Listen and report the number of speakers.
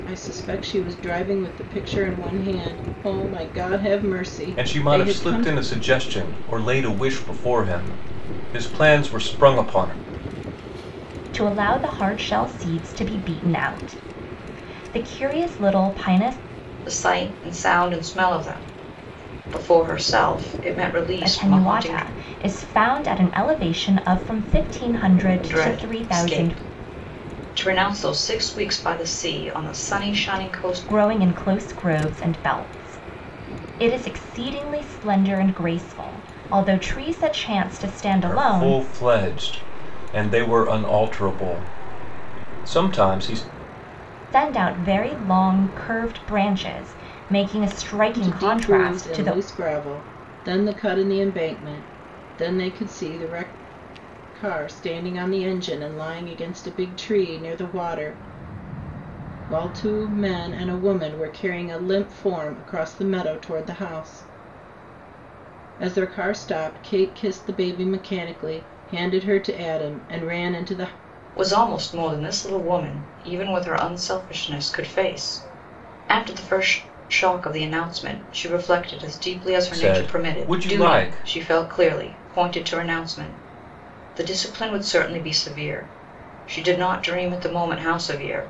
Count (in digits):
4